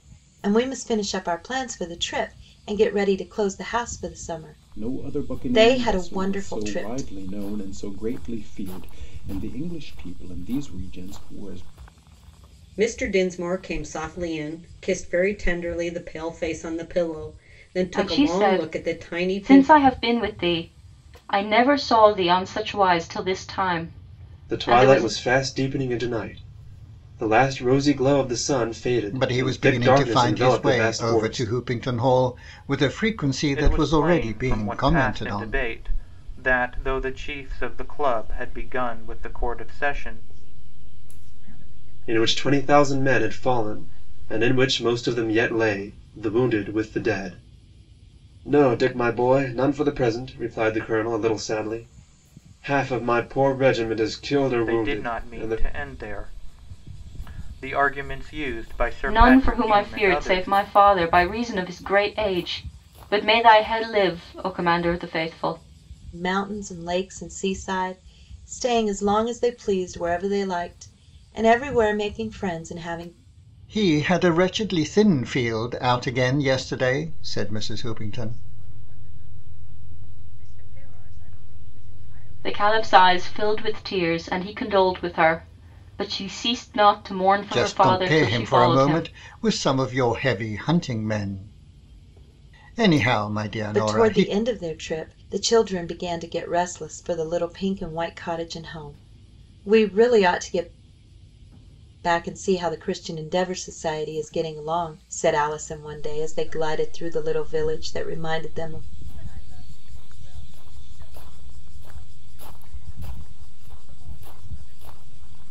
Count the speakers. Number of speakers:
eight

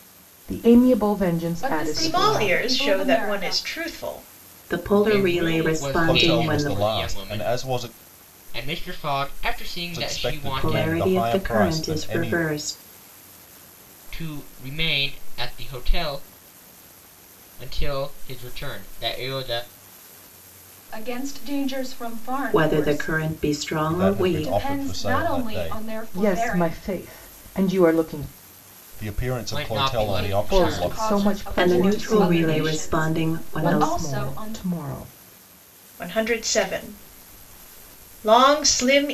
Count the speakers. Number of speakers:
six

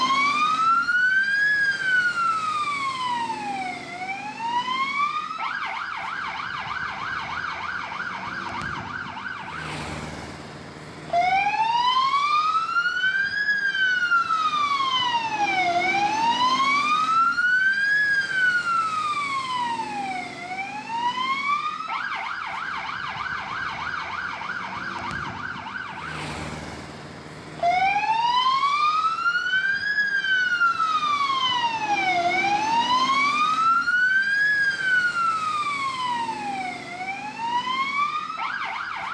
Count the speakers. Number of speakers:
zero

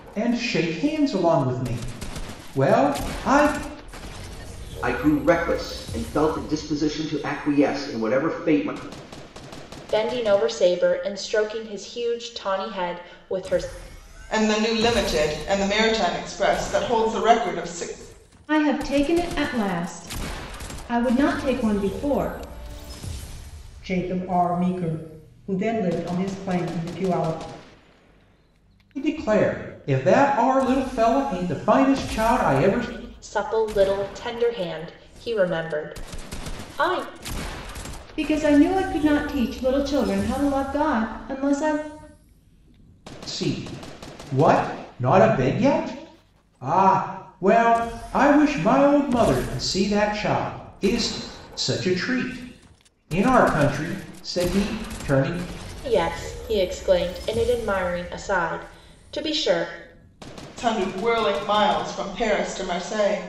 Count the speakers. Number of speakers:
six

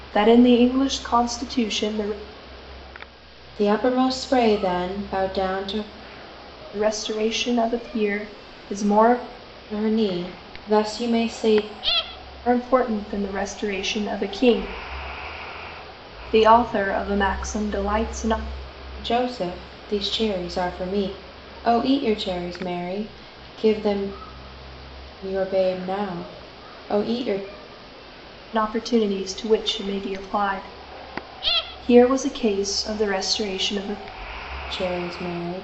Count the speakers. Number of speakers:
two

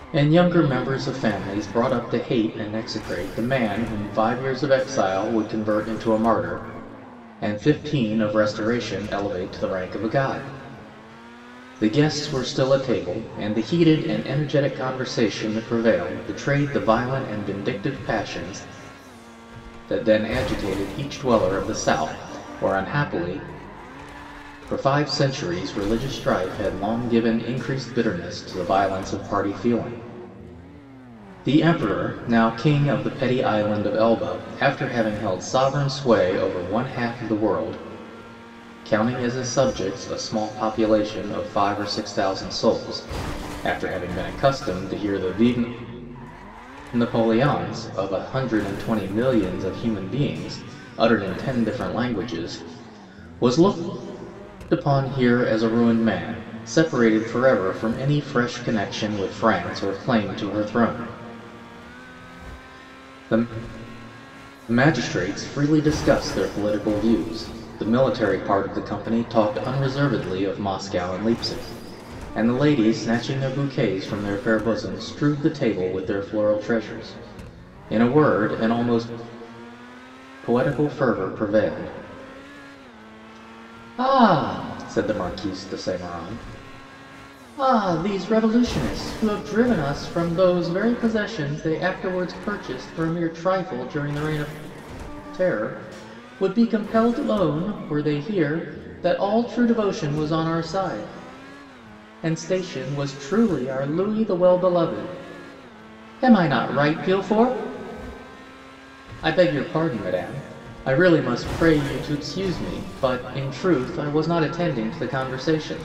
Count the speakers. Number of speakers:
one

